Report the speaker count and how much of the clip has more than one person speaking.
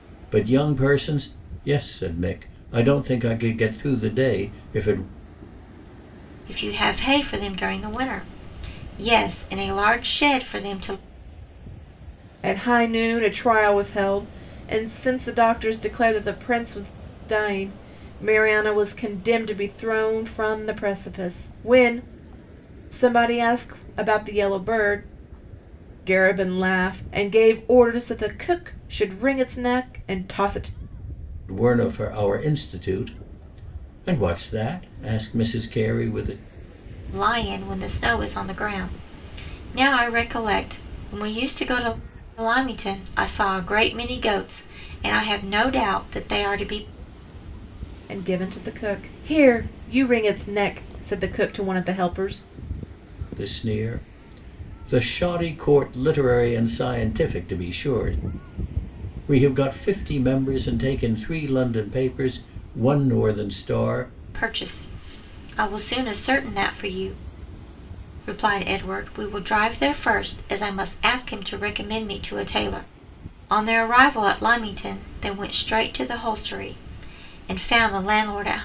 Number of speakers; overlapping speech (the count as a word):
three, no overlap